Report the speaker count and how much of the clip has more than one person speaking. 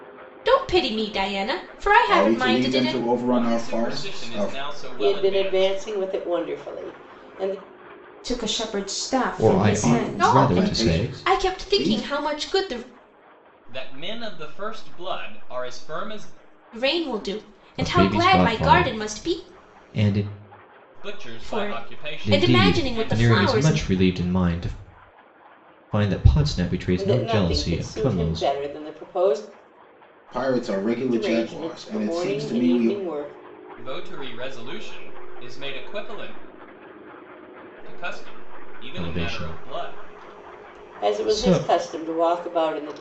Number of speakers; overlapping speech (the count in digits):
6, about 36%